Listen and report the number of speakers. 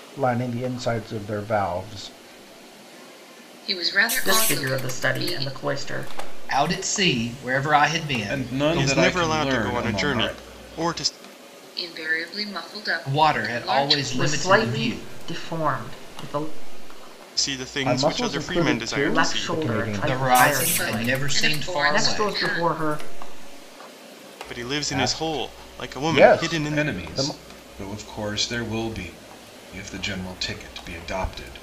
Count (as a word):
six